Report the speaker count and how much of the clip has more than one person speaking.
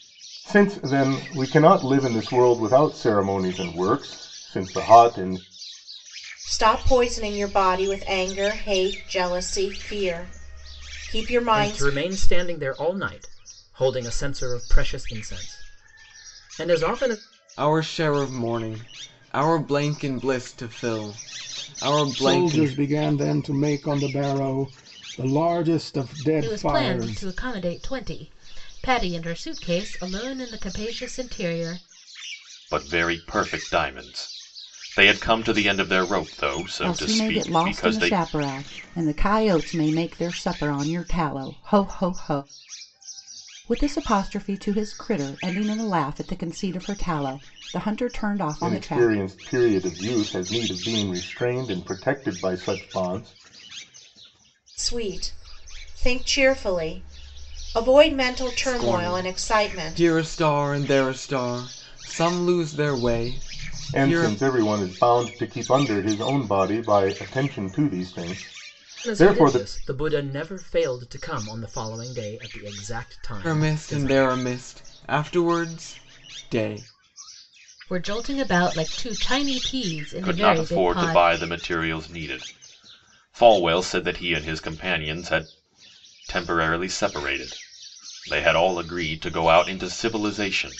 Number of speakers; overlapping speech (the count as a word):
eight, about 9%